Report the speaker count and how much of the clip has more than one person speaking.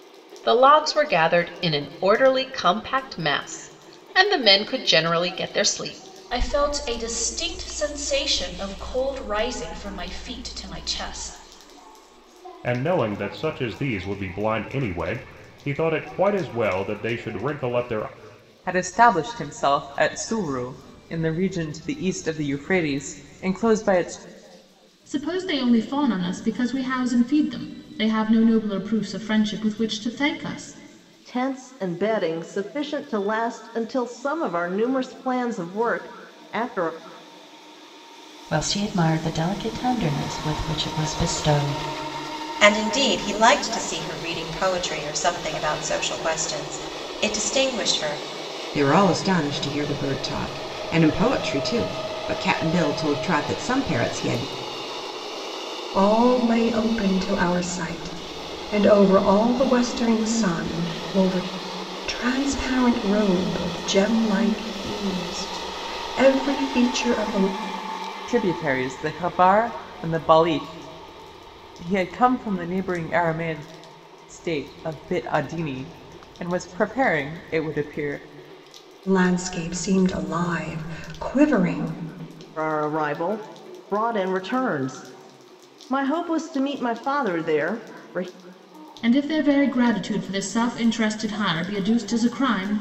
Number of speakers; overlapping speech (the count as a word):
ten, no overlap